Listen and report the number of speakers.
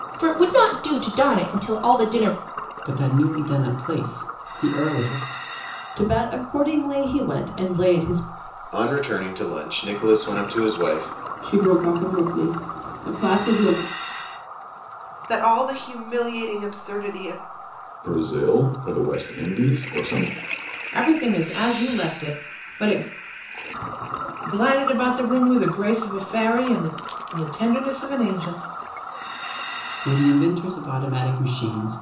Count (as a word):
eight